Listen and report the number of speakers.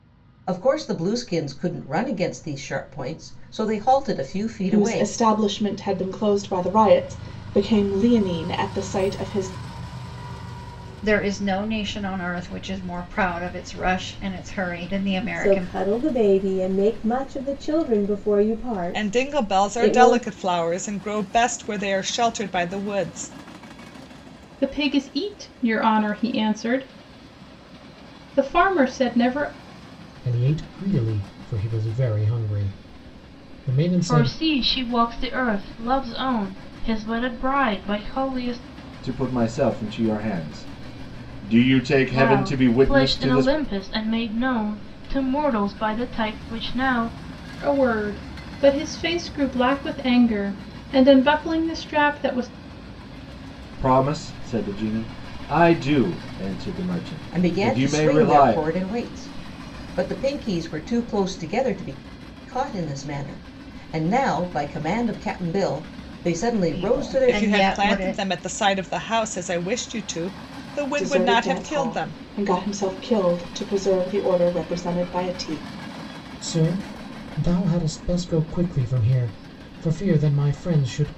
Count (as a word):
nine